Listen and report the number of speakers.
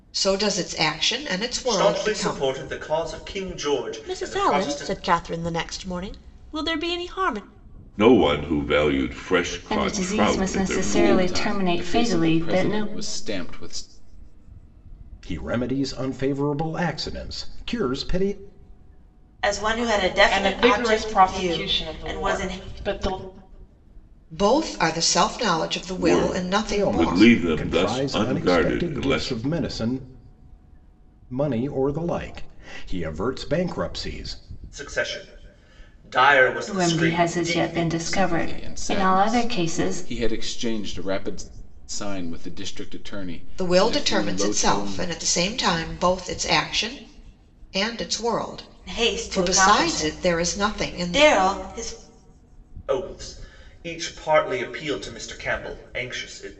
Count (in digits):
9